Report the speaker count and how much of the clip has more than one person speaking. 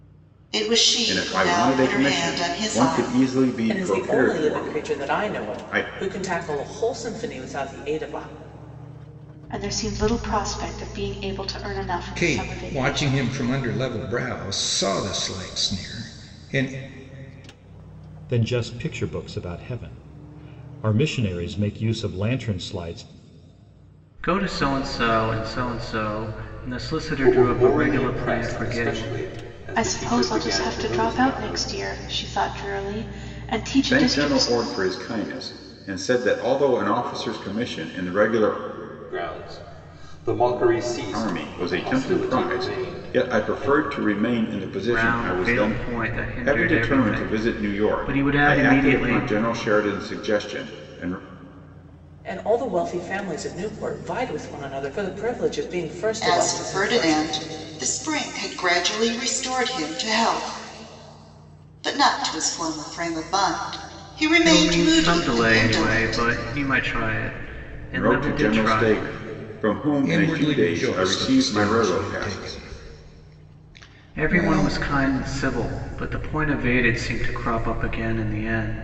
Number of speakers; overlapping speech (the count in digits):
8, about 30%